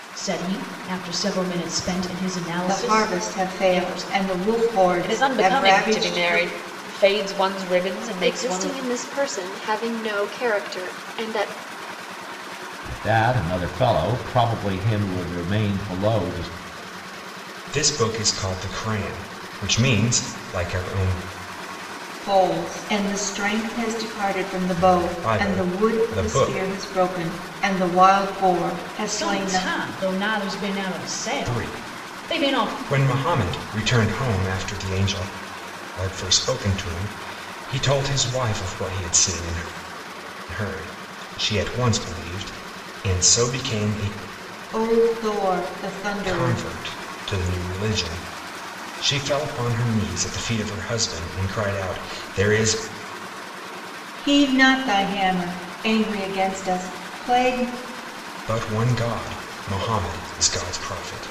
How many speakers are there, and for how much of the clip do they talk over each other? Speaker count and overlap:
6, about 13%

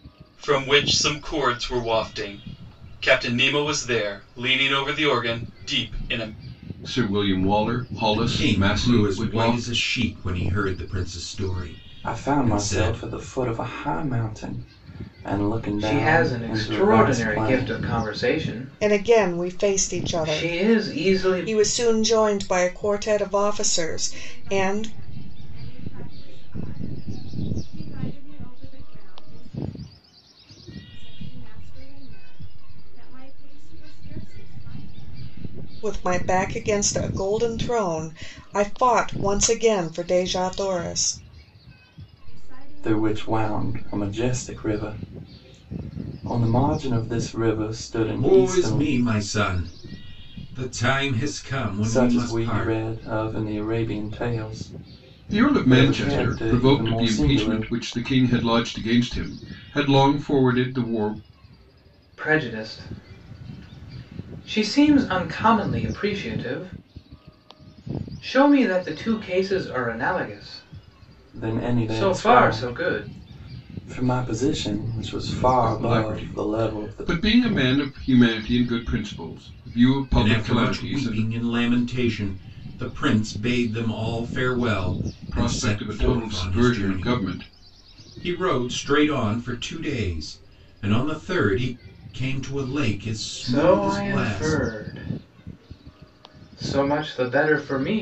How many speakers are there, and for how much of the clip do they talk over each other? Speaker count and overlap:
7, about 24%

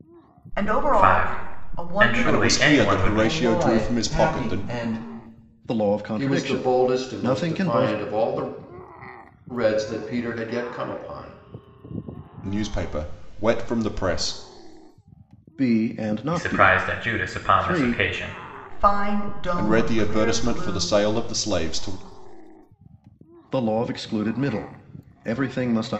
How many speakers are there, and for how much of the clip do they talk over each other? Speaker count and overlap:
6, about 34%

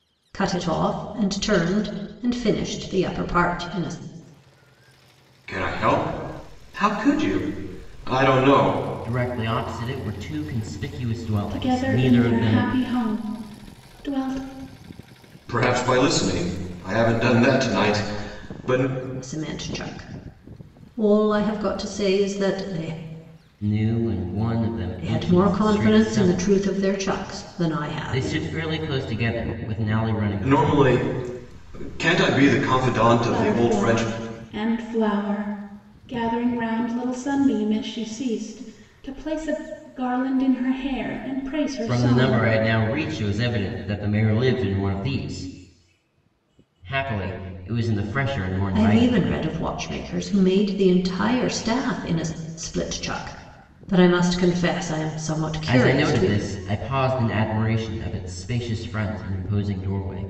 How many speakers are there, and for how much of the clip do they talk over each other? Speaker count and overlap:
4, about 11%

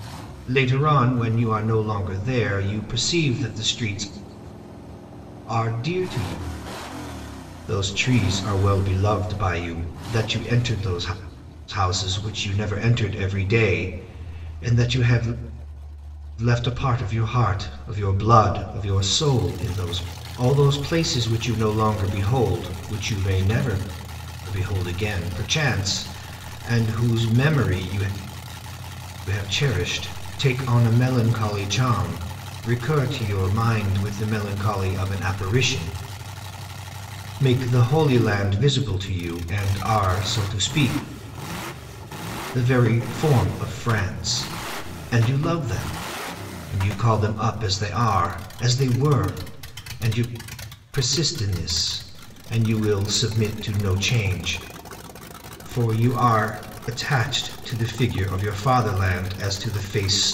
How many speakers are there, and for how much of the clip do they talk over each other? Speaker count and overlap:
1, no overlap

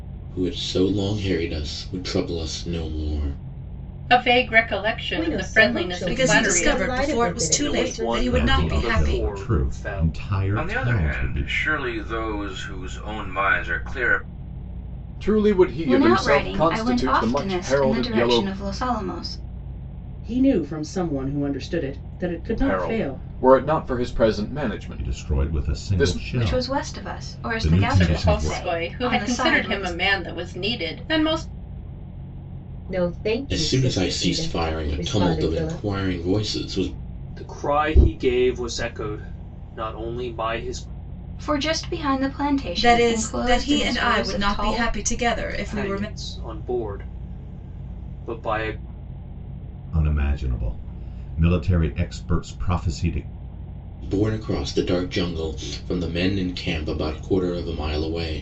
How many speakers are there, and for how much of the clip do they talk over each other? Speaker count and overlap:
10, about 35%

